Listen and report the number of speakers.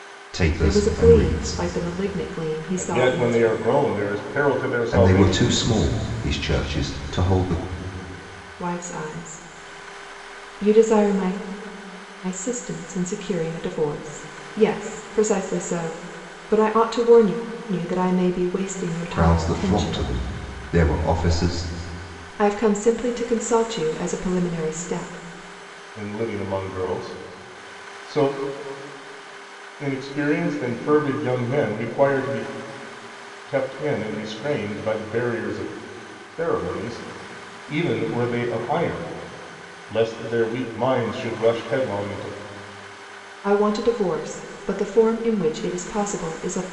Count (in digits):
3